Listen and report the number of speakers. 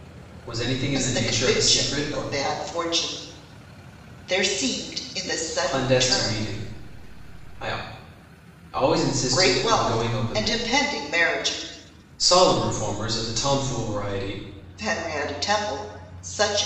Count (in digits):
2